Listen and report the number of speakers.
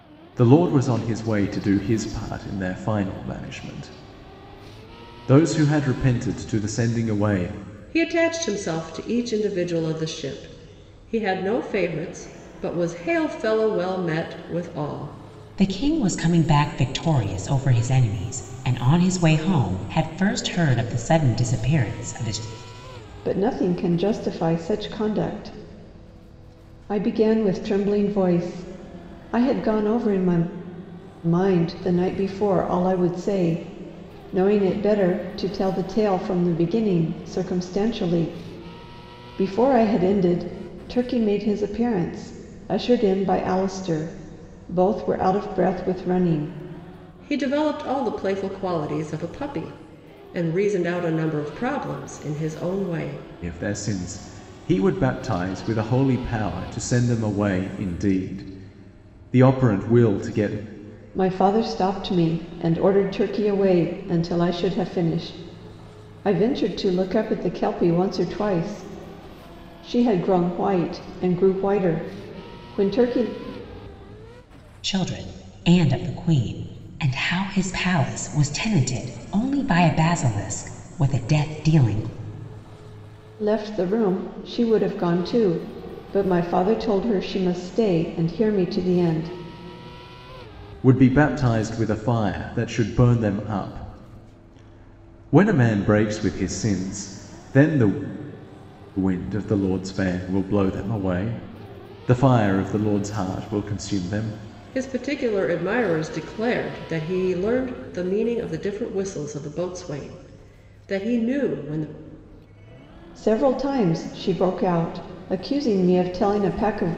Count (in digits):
4